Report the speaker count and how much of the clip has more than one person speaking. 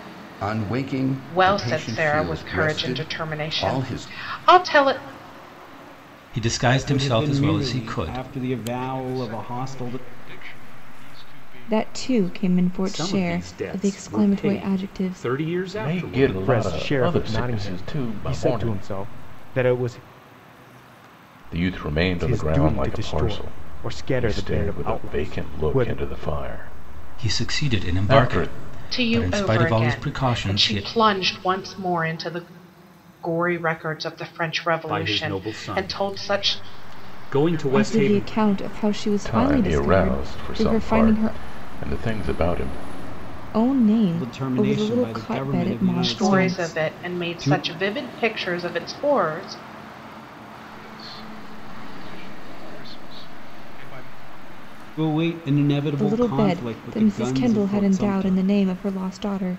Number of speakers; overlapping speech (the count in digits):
9, about 53%